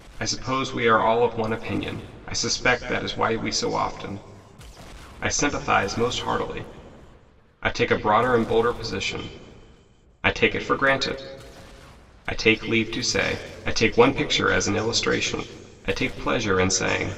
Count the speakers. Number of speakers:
one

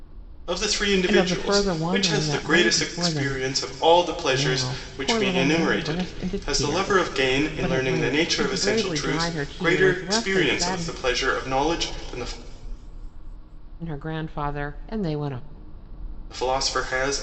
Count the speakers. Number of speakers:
two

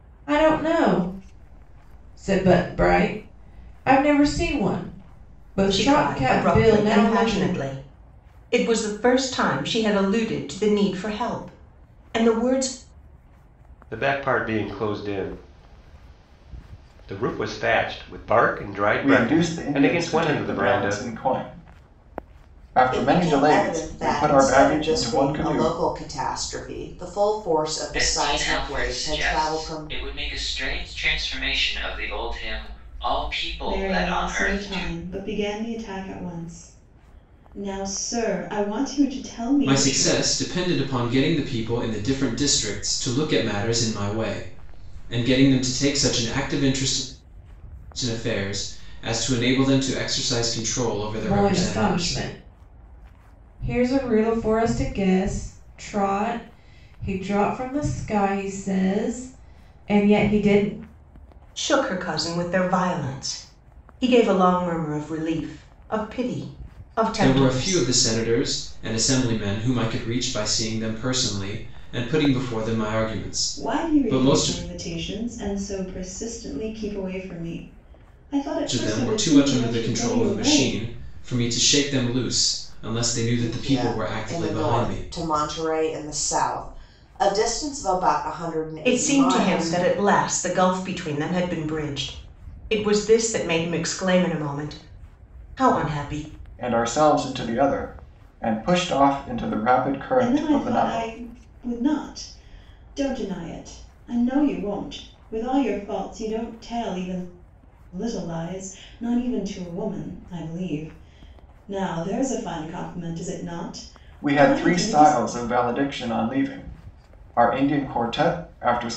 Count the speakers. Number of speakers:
eight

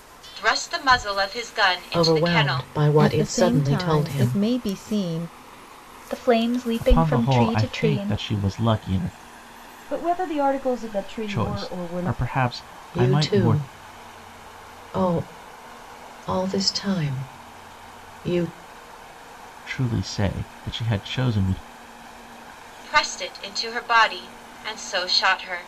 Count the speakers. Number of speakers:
six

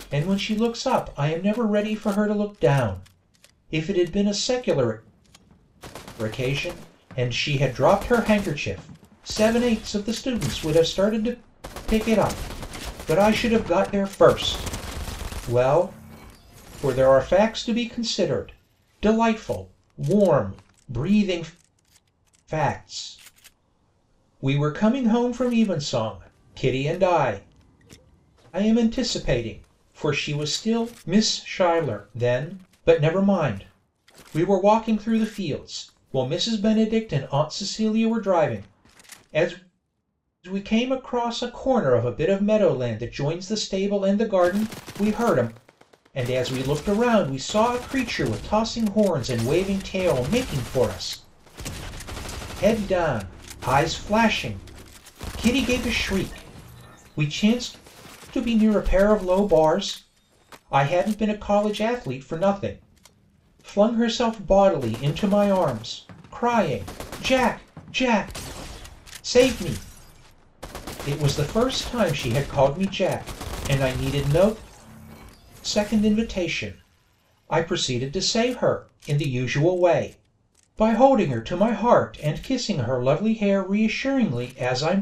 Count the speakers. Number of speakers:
one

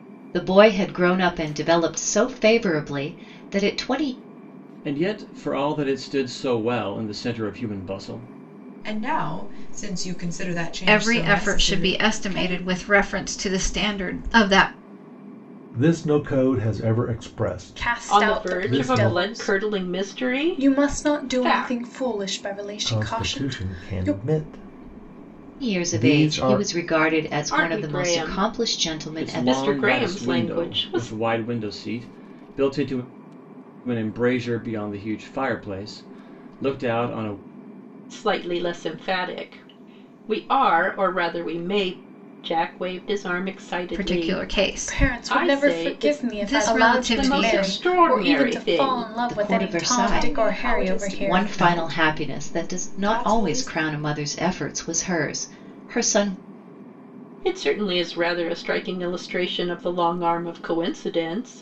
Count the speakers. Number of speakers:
seven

